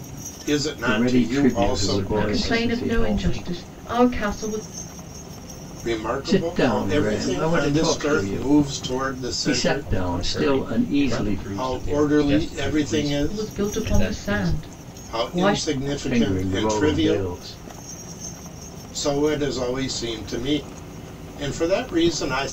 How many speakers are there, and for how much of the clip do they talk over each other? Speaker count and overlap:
4, about 54%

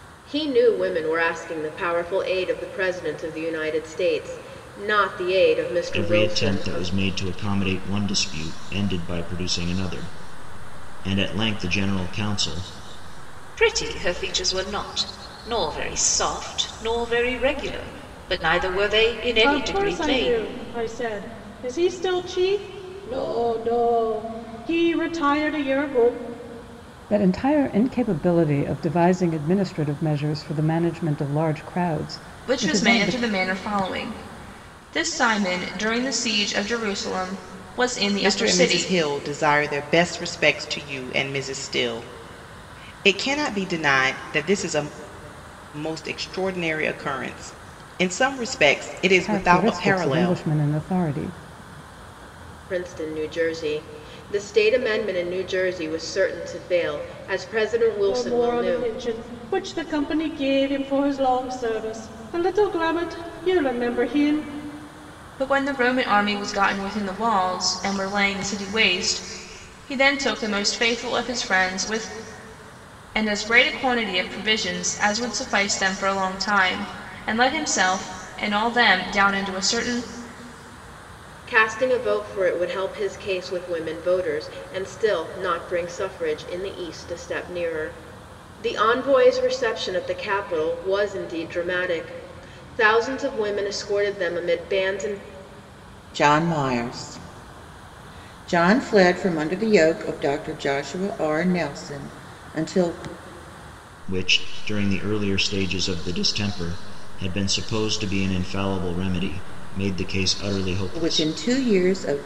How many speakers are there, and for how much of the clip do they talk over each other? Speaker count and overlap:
7, about 5%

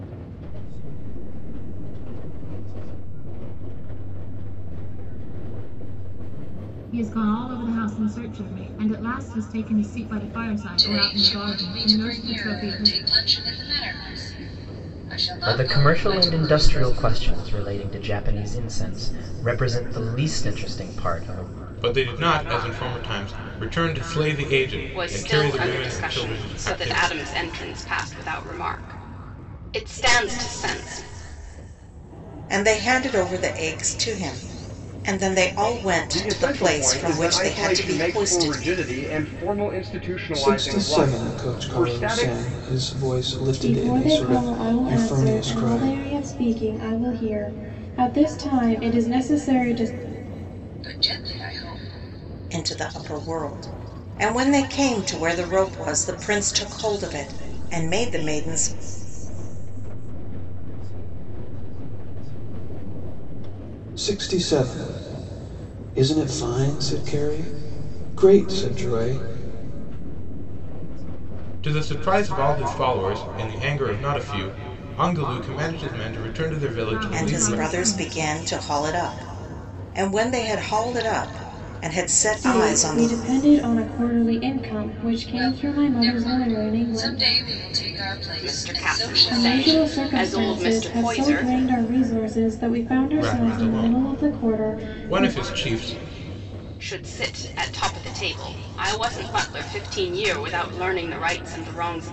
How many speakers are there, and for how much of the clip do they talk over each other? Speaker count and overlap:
10, about 27%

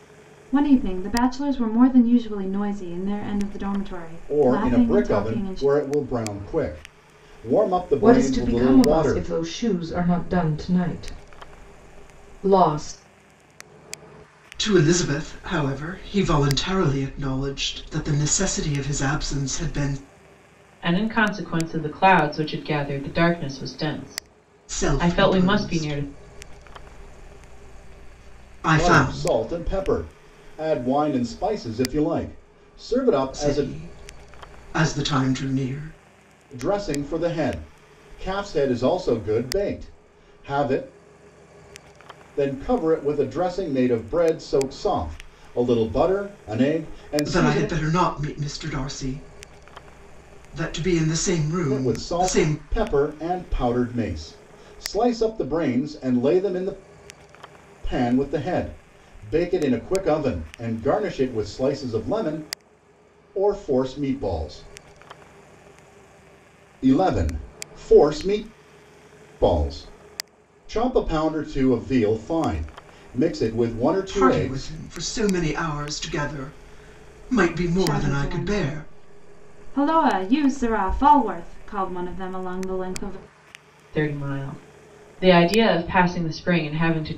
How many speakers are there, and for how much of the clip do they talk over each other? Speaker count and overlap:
5, about 10%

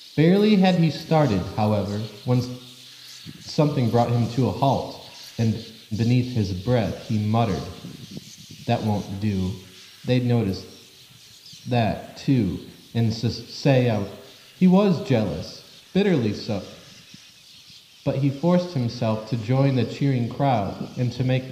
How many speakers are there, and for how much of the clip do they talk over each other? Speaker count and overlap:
1, no overlap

